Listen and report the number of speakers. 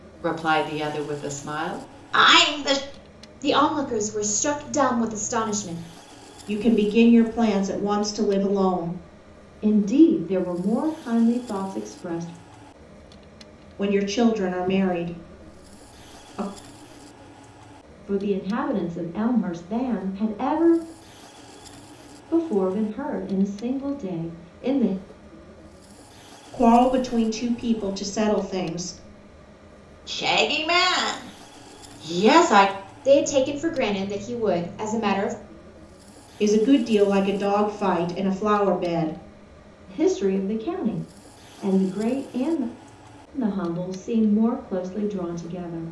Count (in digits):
4